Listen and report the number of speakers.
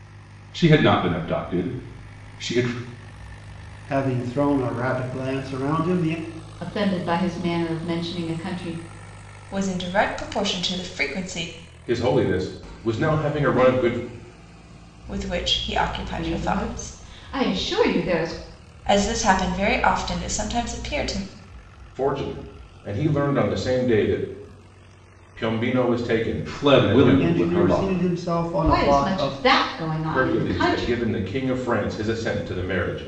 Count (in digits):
5